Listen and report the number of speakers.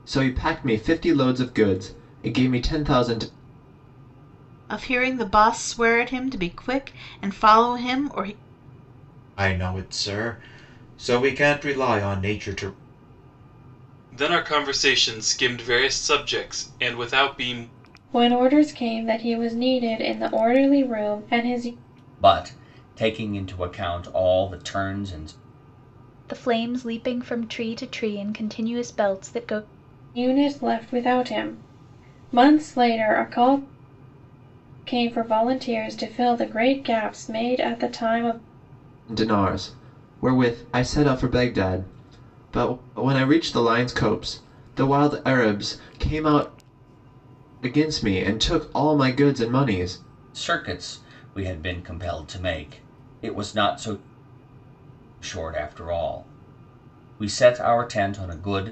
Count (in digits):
7